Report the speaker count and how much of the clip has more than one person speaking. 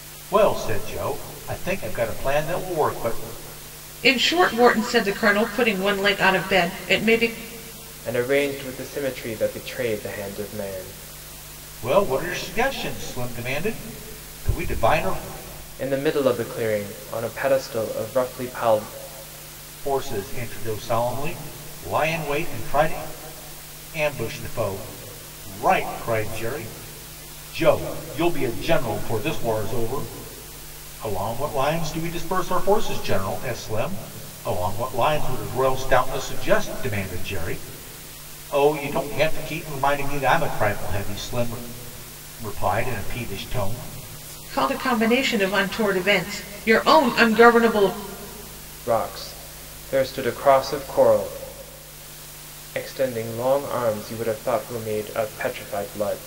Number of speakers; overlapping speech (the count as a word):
three, no overlap